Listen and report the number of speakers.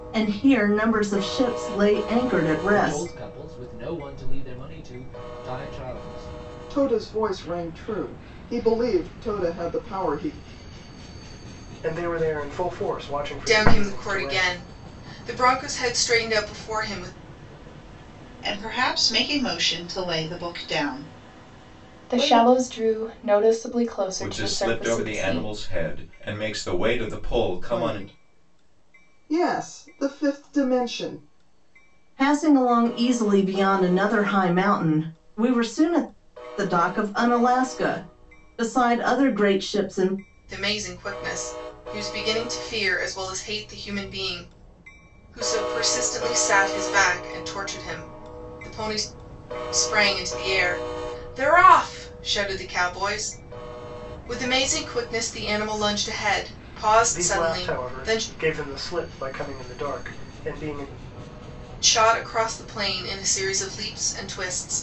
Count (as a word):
eight